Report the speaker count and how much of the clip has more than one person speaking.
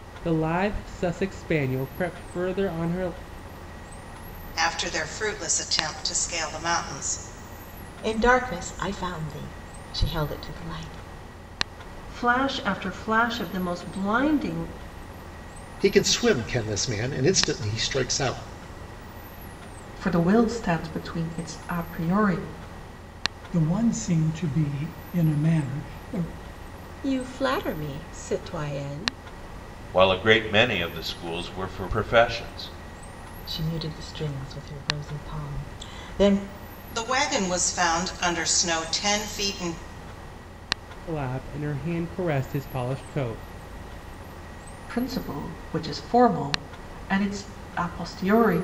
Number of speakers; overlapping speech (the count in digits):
9, no overlap